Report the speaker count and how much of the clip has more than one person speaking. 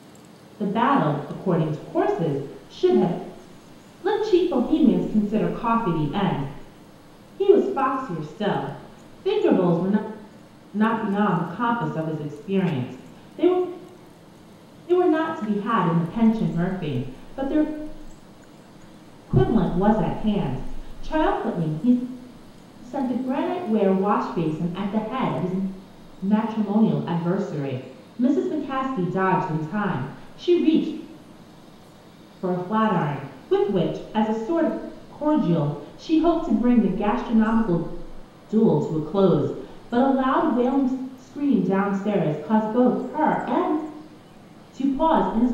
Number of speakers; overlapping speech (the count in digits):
1, no overlap